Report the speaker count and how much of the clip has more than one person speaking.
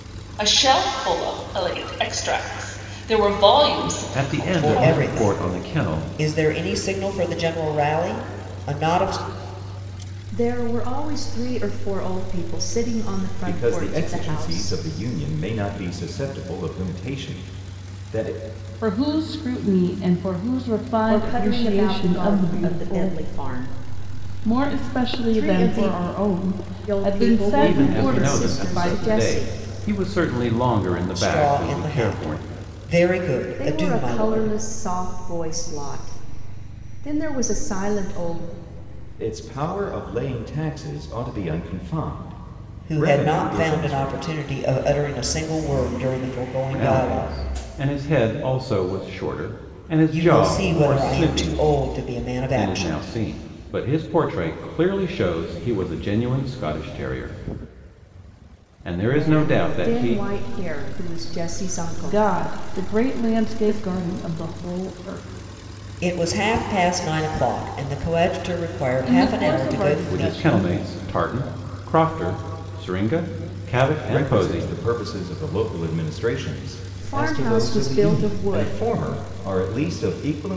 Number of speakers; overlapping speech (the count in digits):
6, about 28%